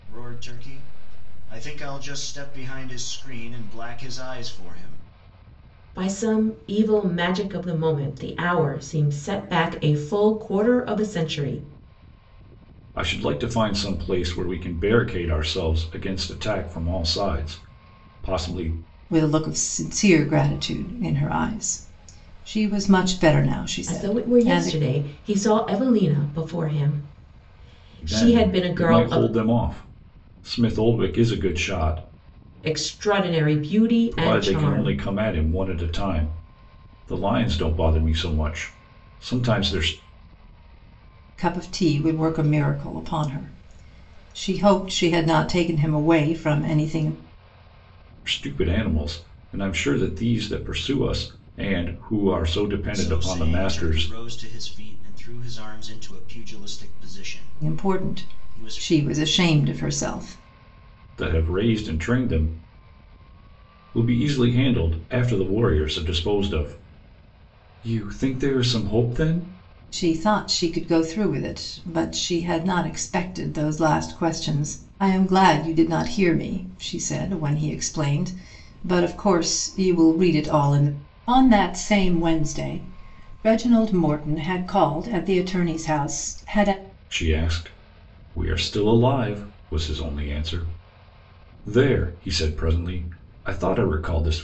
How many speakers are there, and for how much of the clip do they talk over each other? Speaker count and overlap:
4, about 6%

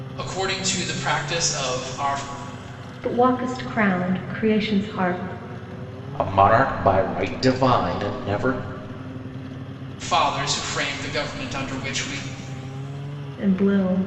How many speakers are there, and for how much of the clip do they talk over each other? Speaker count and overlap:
3, no overlap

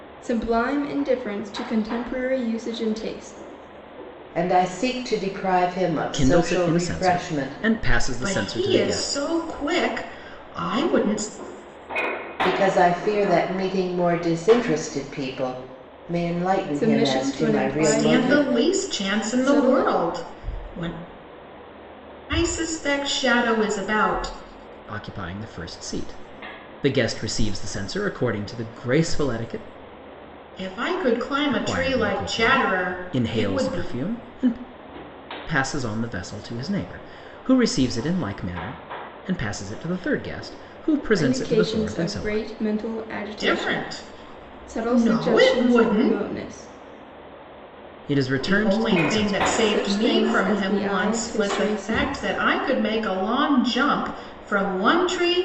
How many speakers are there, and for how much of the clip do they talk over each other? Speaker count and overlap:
4, about 28%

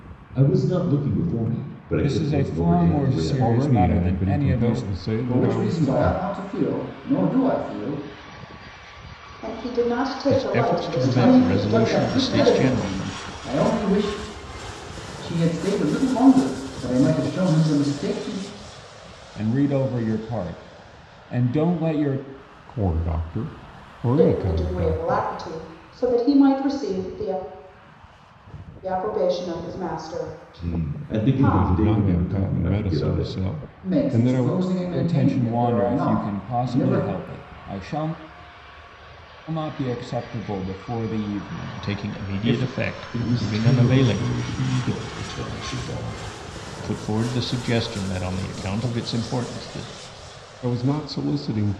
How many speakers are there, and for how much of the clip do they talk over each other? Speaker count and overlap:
6, about 32%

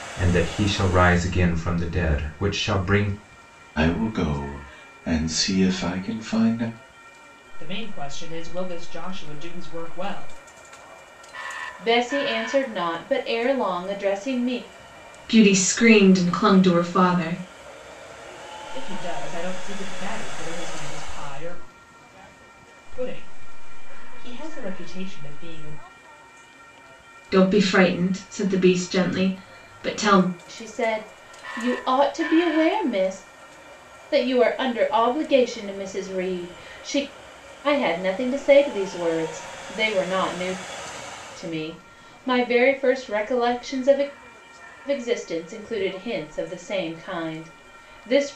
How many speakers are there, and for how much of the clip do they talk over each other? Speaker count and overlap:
5, no overlap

